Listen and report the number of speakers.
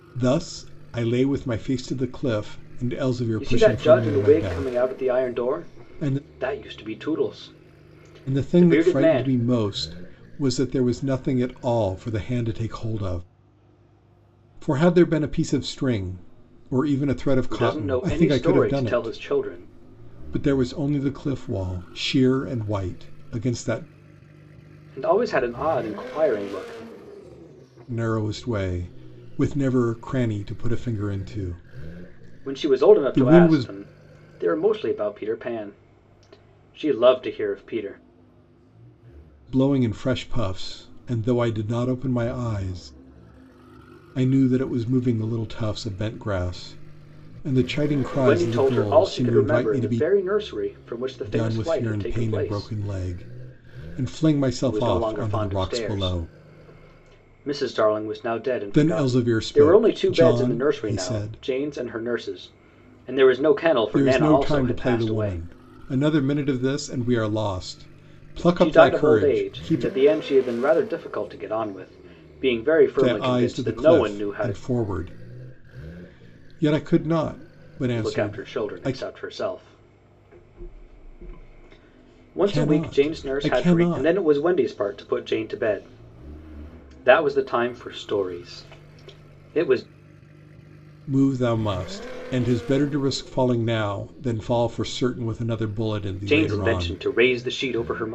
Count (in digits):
2